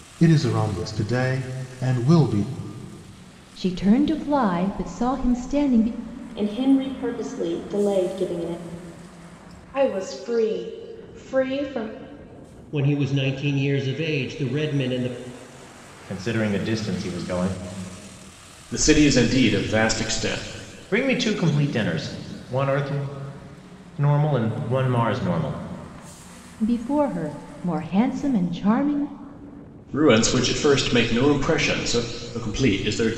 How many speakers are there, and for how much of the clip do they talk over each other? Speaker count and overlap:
7, no overlap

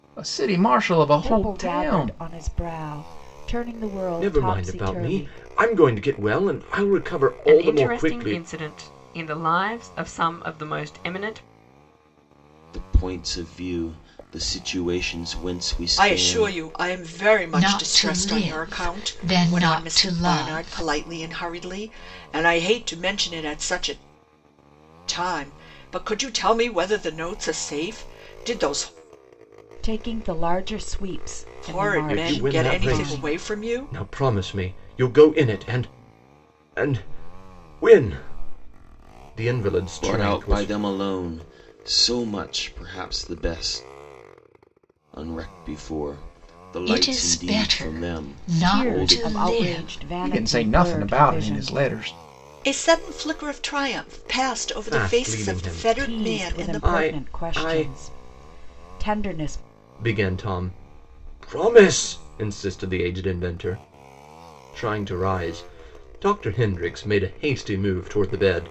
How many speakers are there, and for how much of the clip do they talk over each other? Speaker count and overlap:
7, about 26%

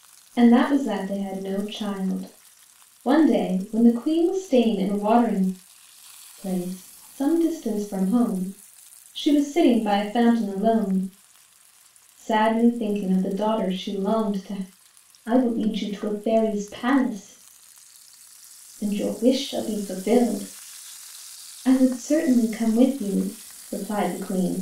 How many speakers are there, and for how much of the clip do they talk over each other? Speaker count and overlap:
1, no overlap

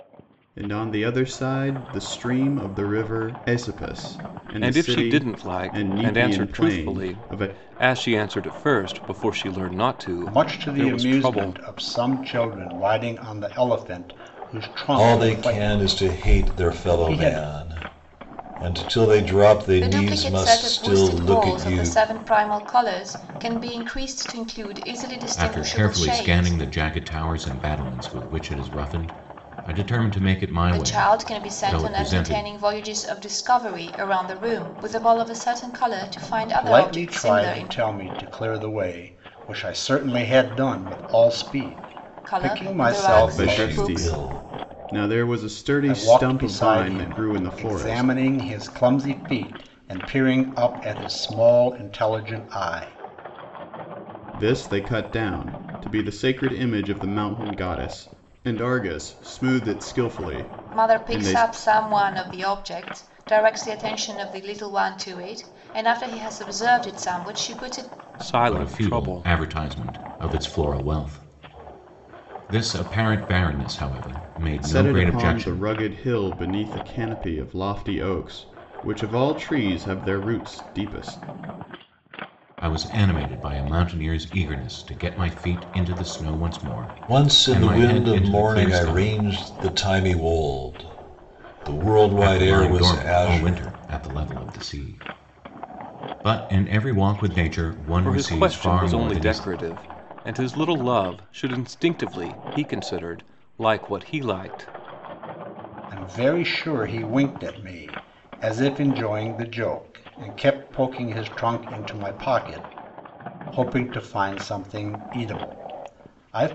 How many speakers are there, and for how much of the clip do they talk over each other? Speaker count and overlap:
6, about 22%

